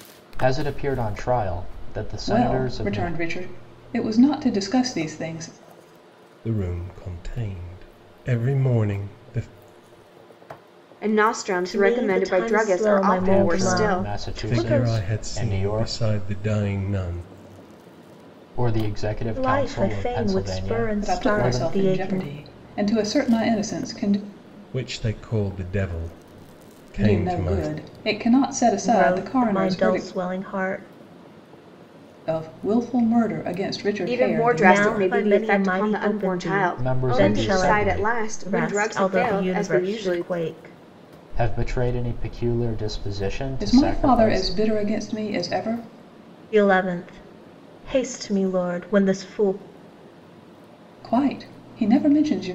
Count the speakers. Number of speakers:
five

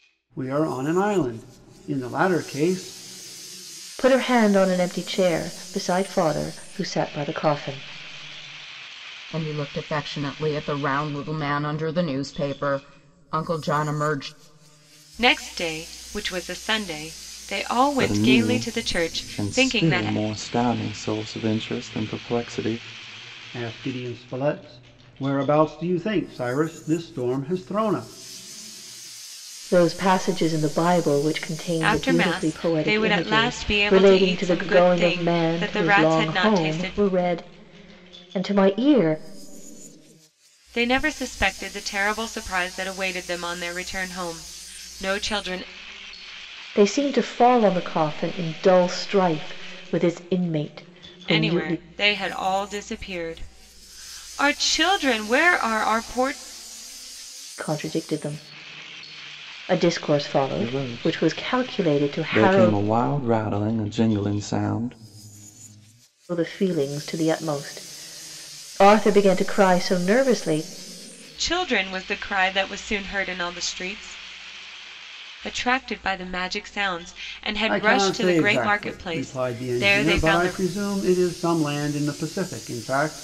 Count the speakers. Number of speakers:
five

